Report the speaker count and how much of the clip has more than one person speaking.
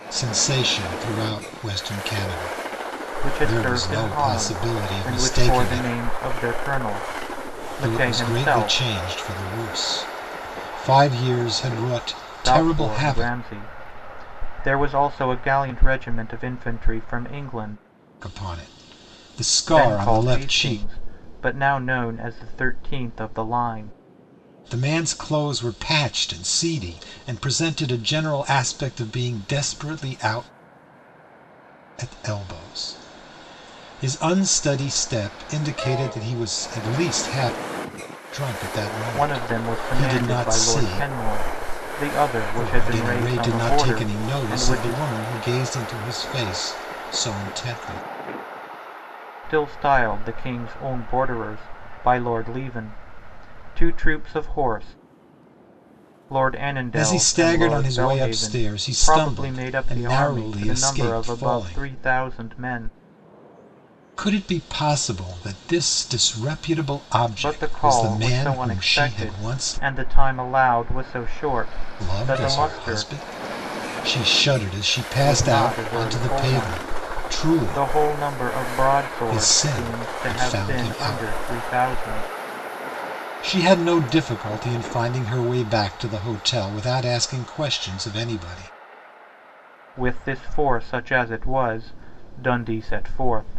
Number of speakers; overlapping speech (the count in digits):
2, about 25%